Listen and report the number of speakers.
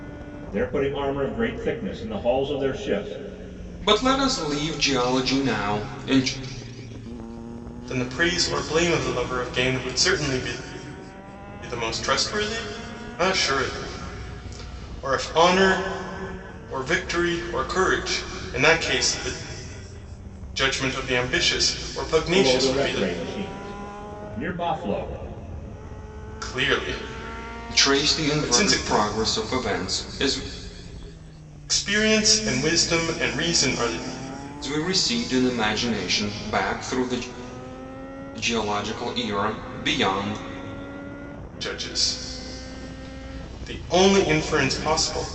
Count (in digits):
3